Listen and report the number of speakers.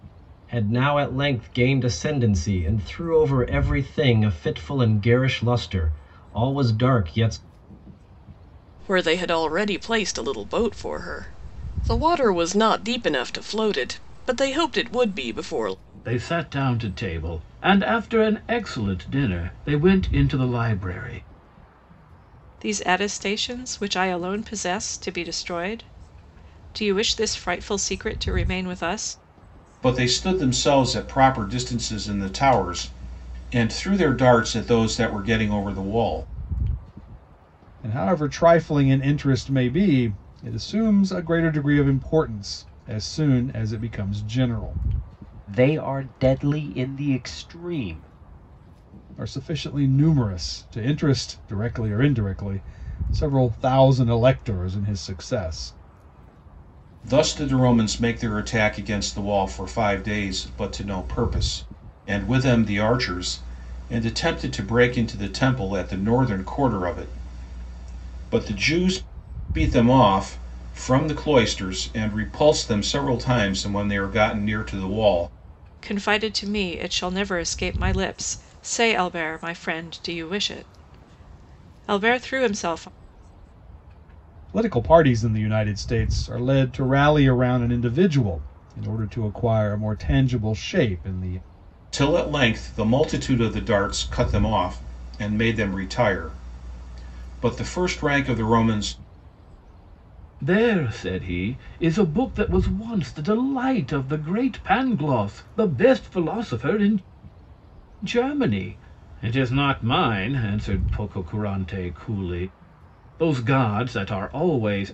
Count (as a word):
seven